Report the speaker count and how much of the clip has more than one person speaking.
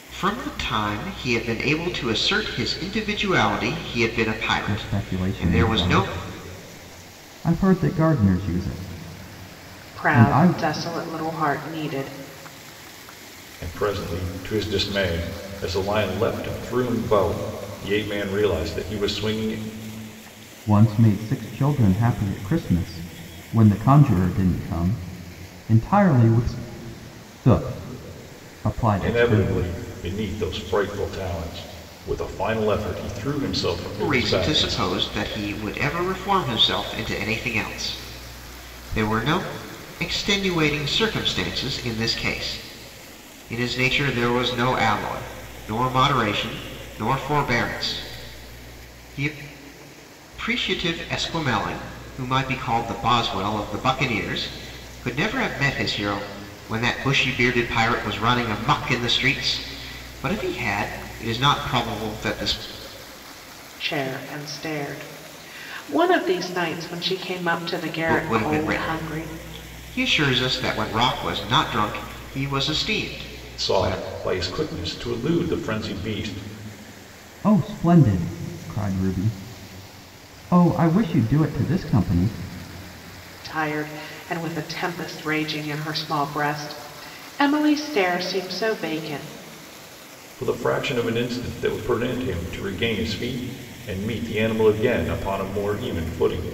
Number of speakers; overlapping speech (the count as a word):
four, about 6%